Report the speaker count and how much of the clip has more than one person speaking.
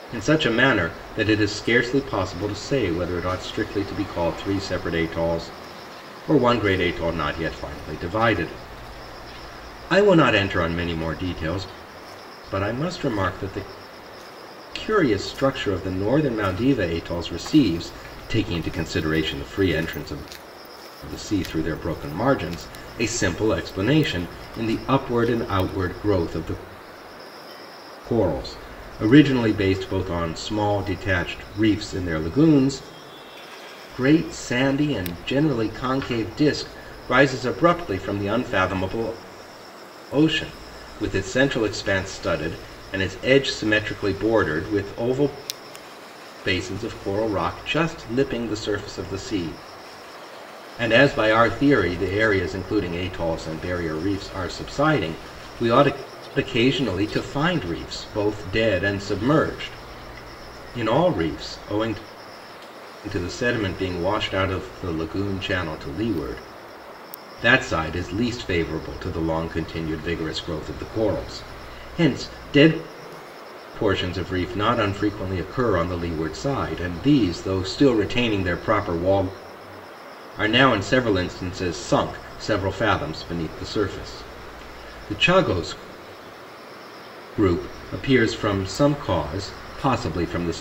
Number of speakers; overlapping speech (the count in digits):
1, no overlap